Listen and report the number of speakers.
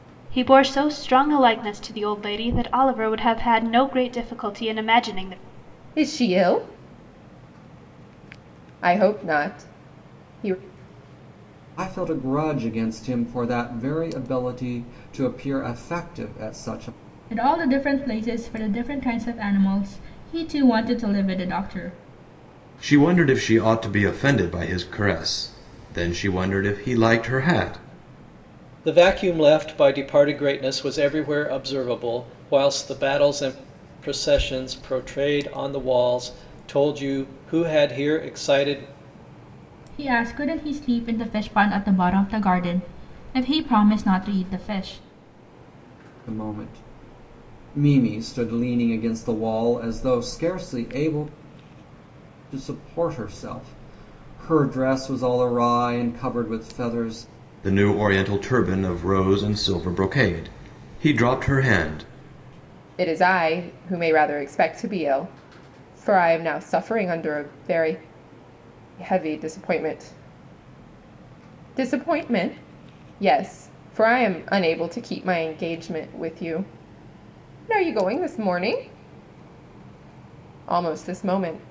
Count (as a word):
six